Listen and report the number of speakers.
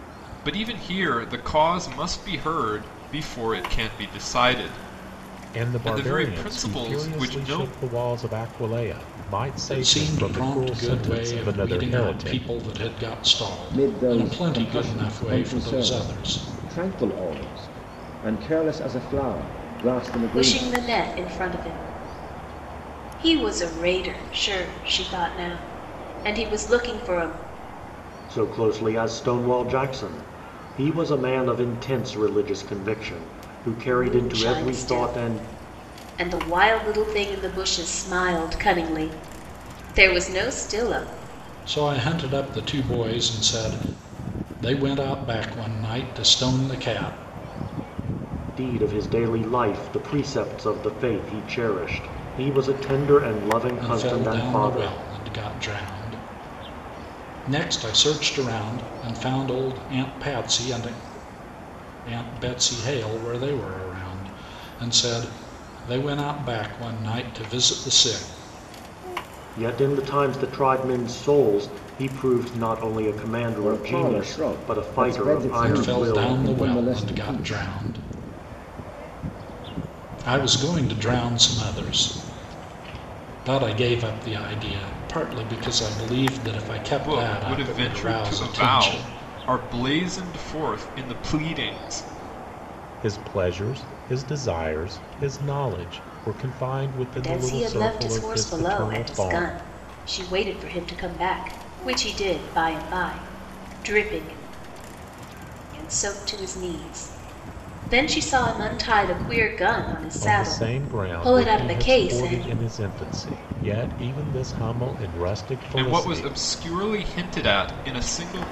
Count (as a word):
six